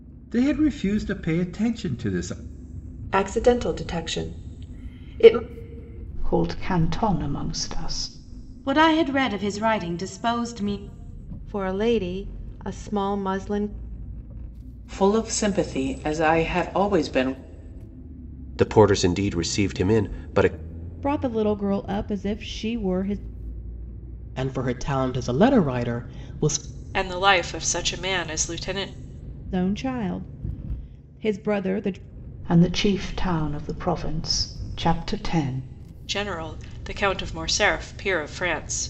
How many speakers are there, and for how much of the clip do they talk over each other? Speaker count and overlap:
ten, no overlap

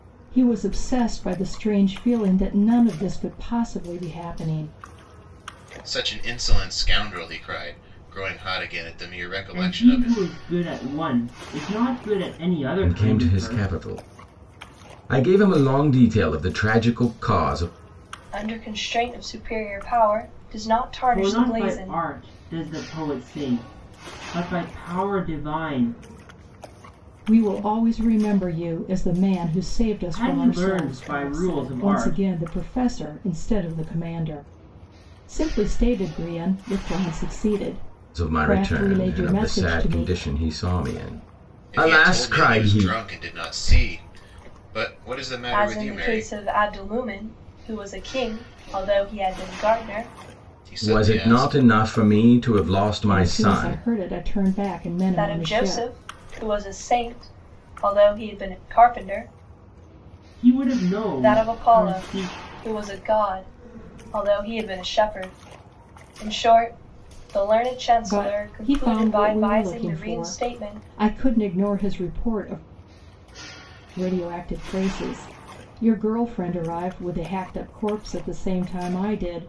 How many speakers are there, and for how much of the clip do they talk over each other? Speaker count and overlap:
five, about 19%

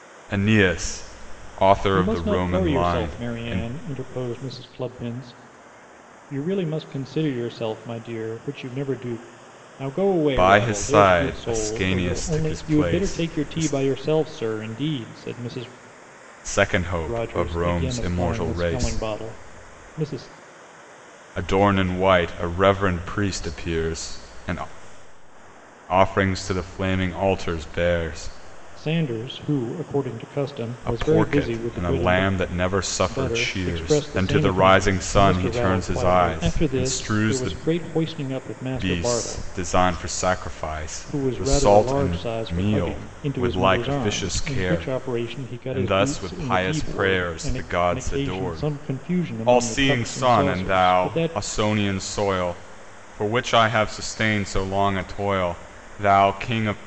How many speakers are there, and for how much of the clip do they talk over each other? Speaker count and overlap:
two, about 39%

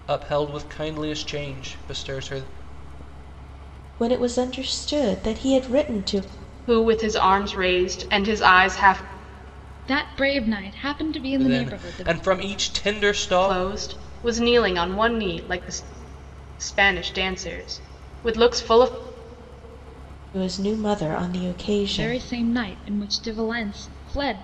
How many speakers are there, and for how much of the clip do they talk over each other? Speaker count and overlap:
four, about 6%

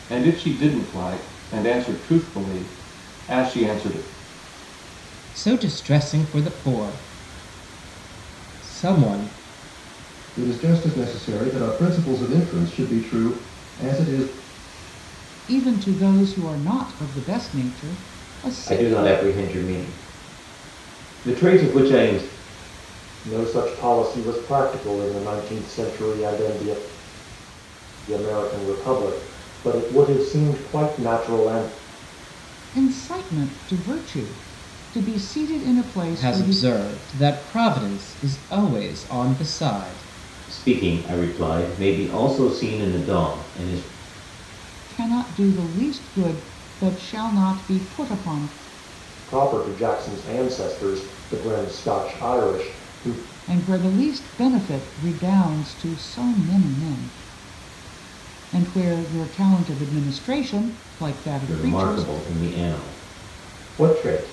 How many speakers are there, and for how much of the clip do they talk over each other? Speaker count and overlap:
six, about 3%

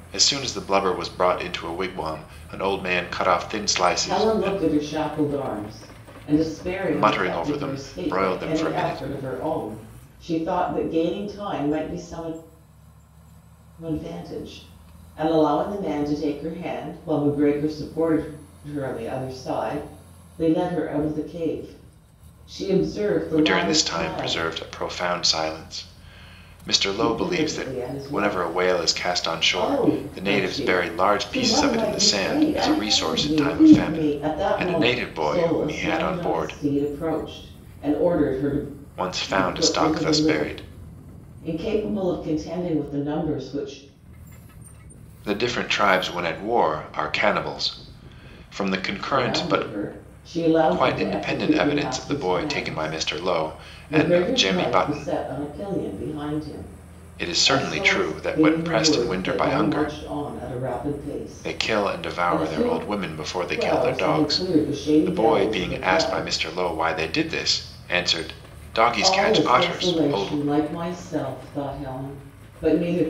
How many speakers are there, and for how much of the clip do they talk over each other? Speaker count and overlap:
two, about 37%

